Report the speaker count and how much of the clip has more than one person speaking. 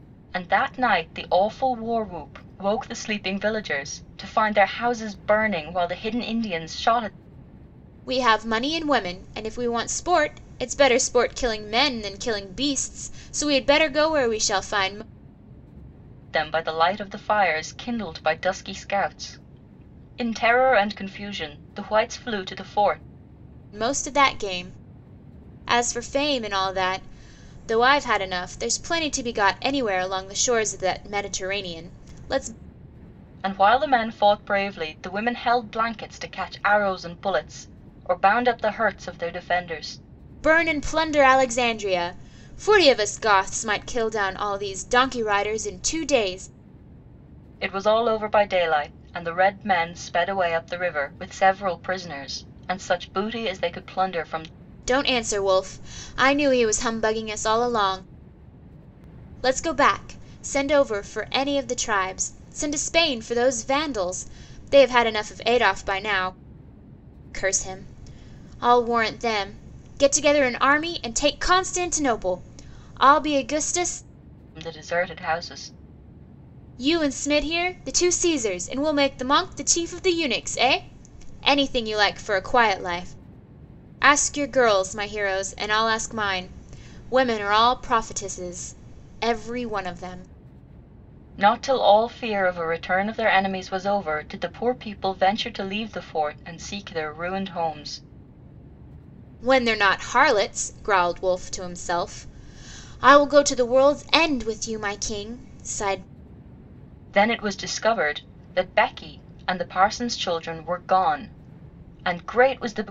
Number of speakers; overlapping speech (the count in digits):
2, no overlap